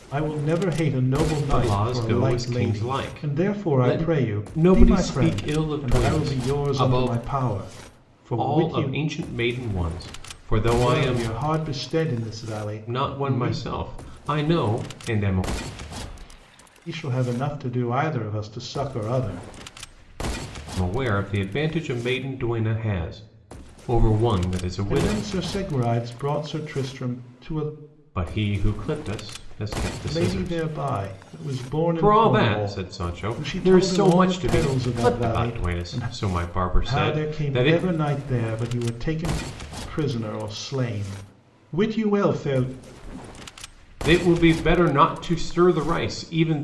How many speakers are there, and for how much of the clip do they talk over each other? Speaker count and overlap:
2, about 26%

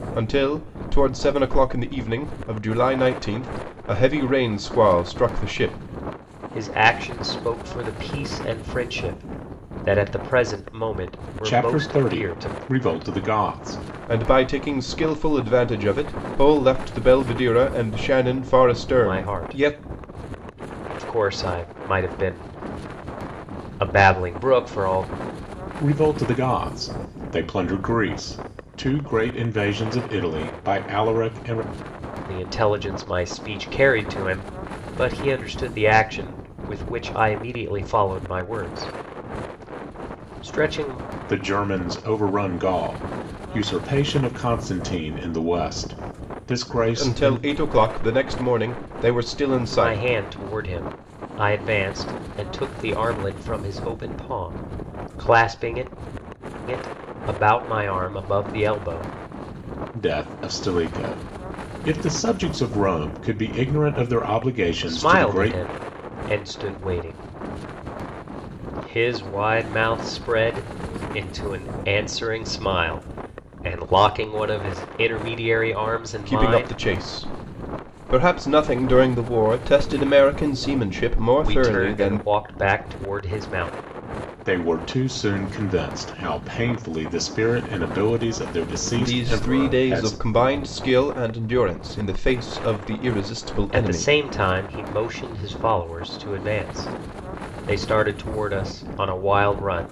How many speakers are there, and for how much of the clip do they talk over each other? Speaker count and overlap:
3, about 7%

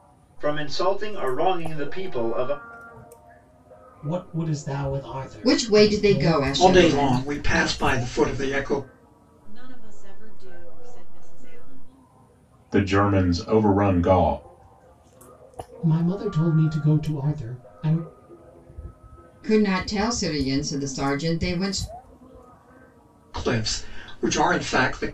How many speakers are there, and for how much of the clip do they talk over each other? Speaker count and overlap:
6, about 9%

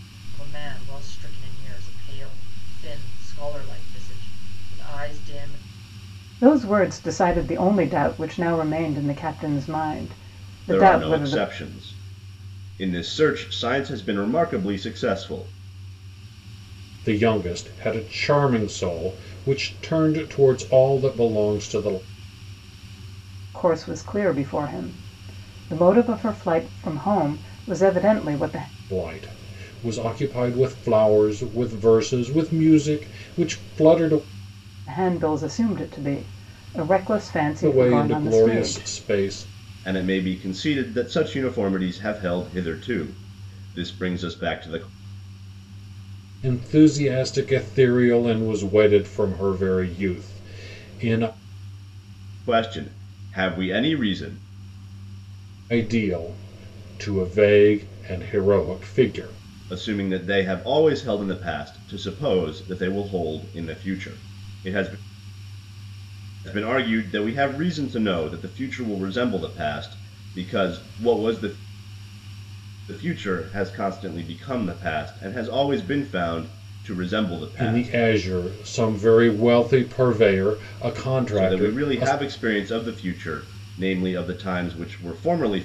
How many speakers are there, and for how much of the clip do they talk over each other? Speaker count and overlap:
4, about 4%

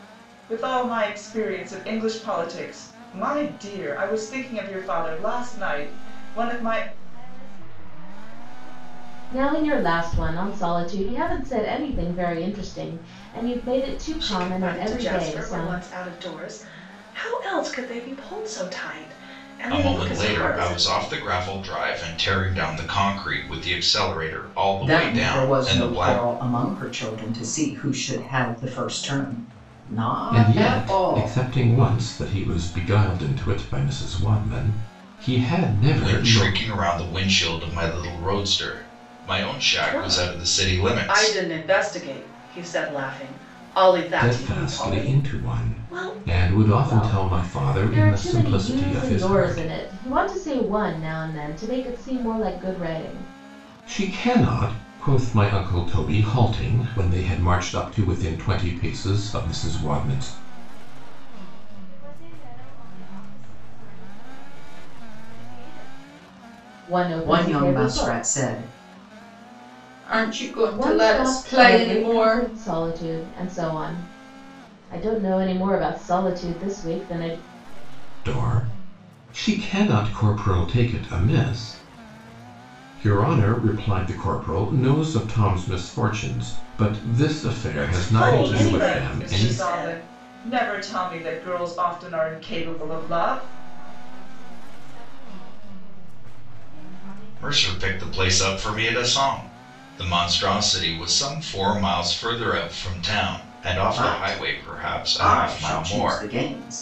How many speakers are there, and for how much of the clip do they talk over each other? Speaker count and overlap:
7, about 26%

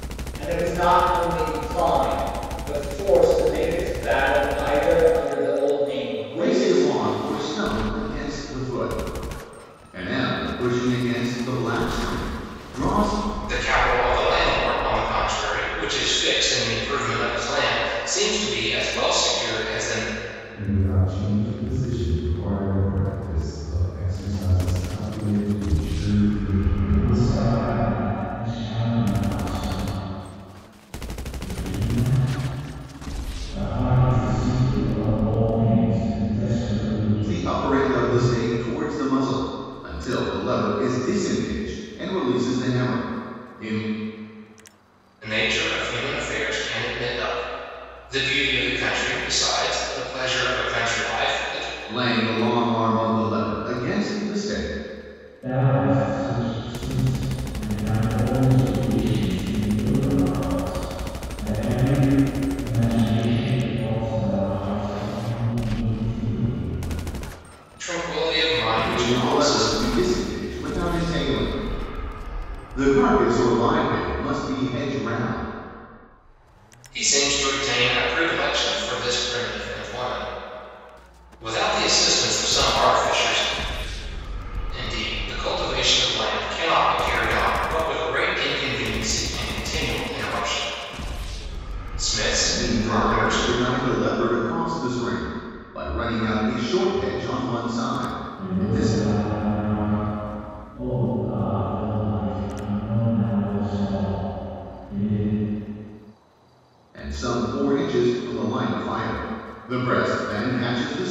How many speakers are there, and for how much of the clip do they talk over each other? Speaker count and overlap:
5, about 4%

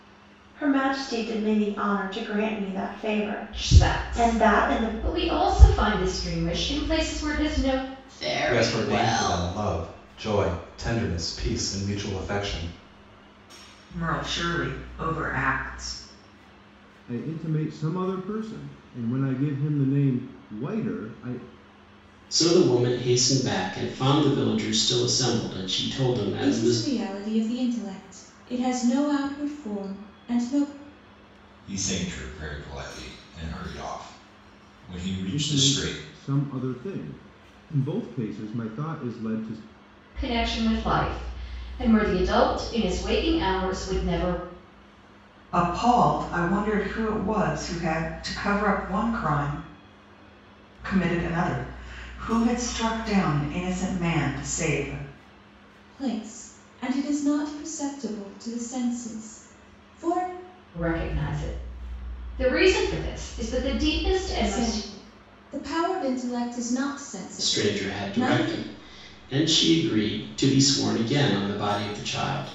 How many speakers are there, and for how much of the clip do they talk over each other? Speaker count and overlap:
9, about 8%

